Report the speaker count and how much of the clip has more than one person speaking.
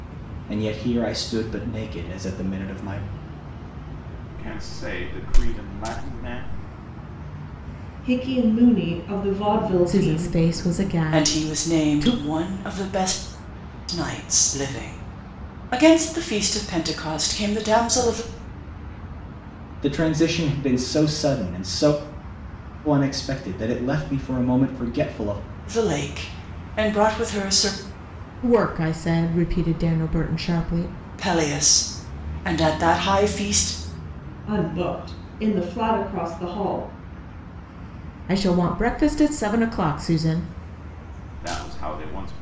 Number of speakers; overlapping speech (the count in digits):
5, about 5%